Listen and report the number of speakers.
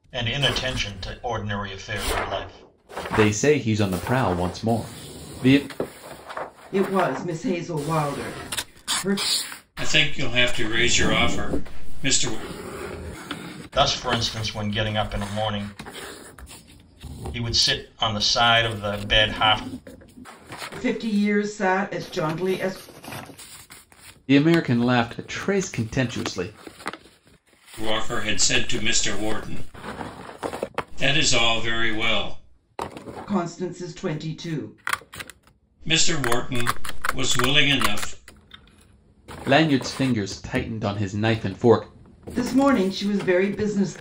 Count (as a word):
four